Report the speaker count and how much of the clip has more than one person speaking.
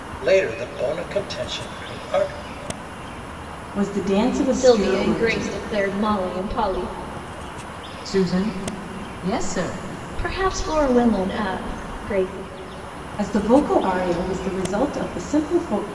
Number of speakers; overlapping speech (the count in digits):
4, about 7%